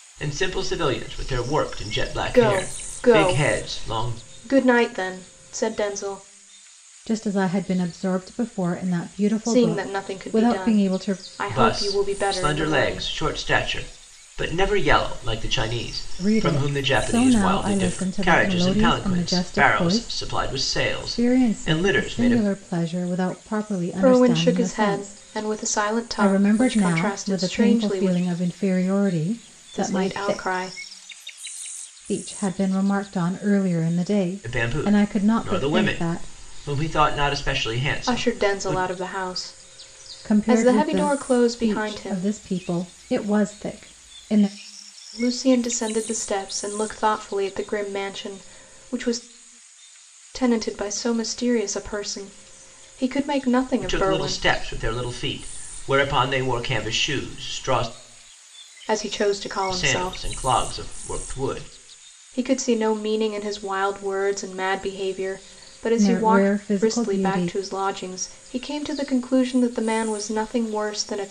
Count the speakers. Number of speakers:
3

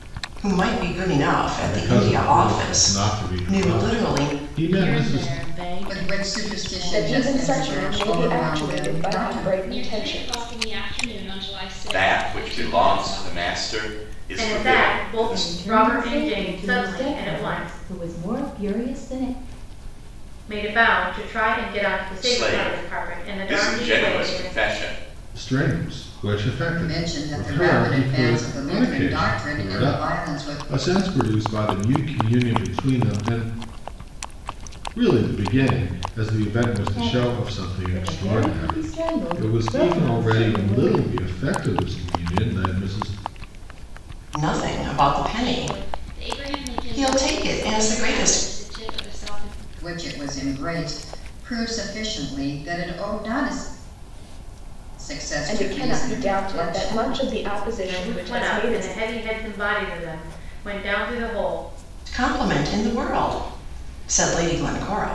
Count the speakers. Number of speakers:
9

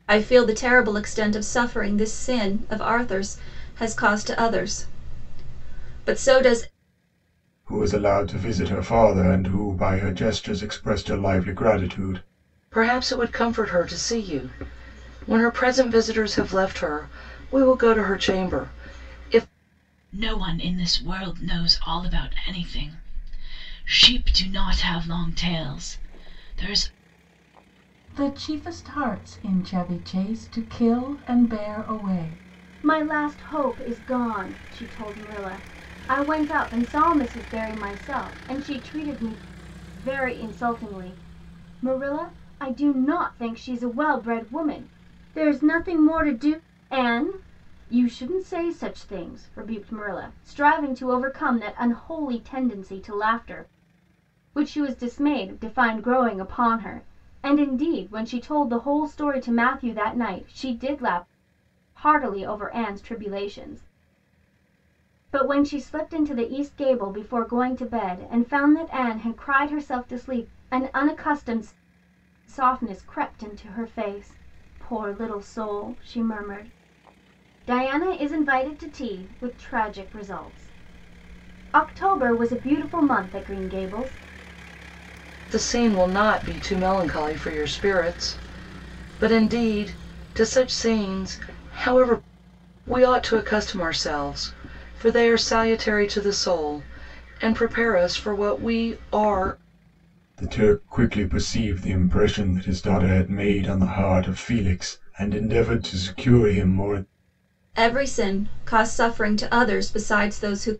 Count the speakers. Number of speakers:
6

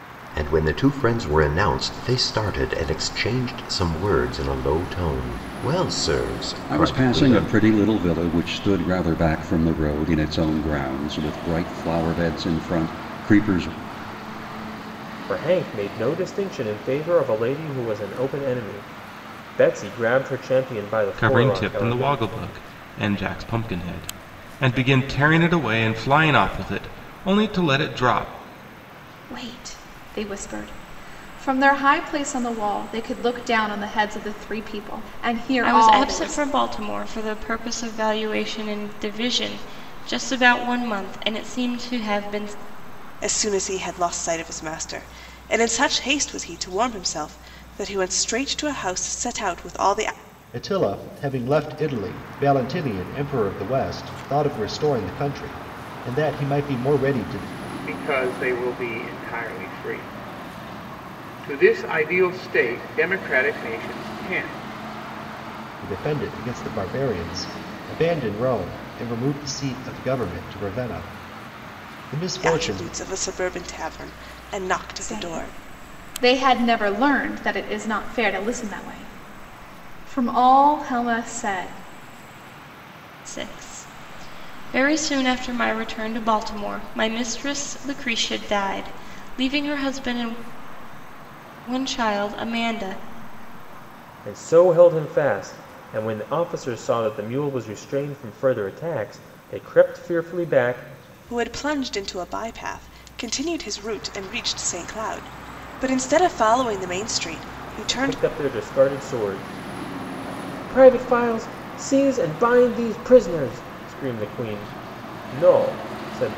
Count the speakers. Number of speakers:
9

